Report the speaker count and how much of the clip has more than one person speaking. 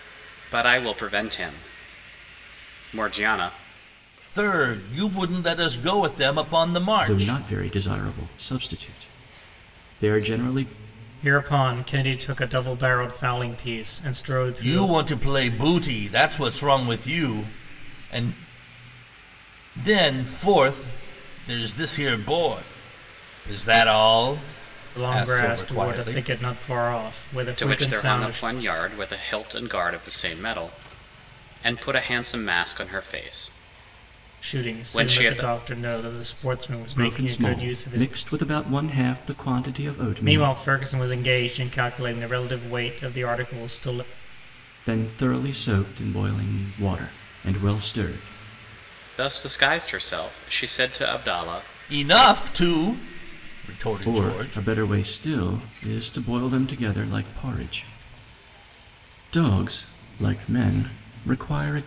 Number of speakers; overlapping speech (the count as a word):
four, about 10%